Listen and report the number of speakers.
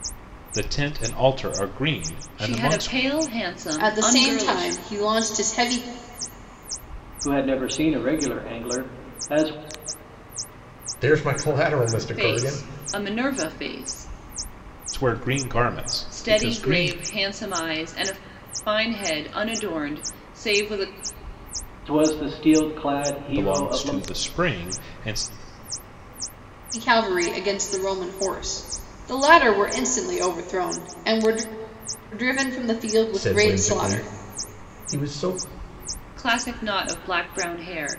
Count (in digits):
5